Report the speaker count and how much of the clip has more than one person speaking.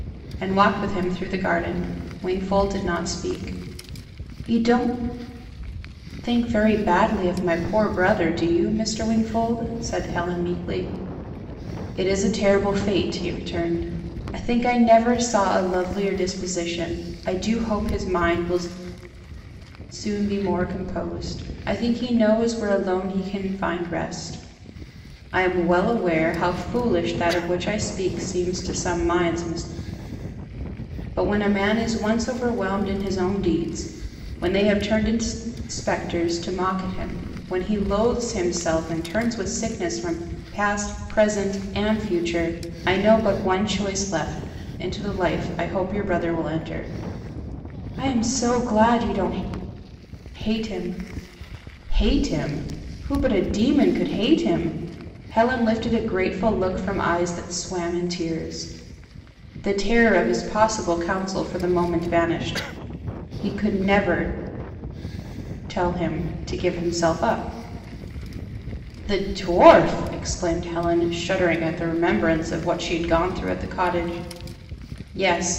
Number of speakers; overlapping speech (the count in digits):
1, no overlap